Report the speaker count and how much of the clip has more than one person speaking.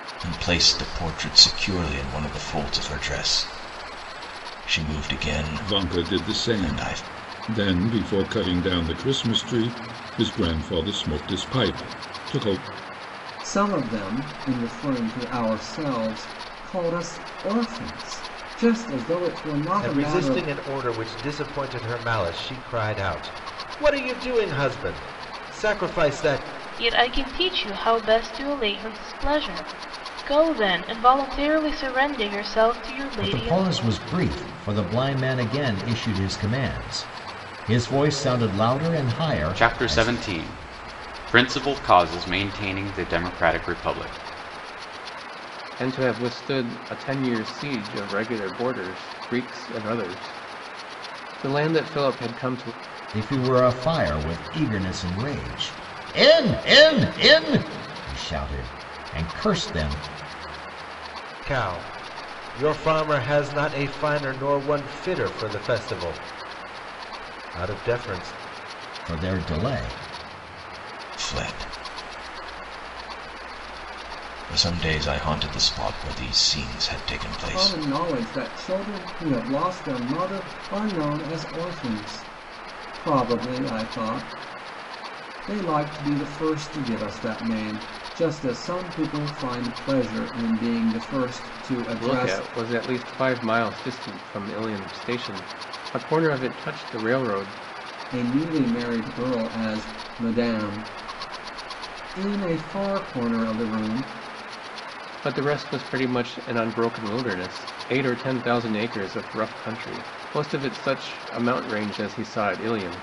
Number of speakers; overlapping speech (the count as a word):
eight, about 4%